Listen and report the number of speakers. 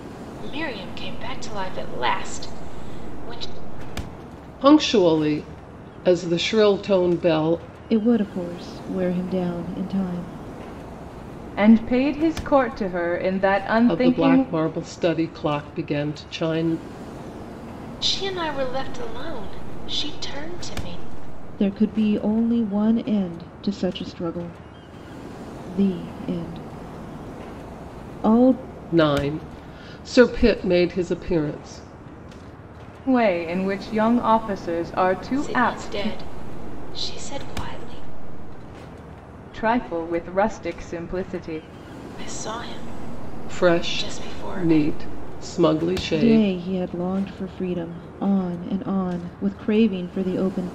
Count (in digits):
4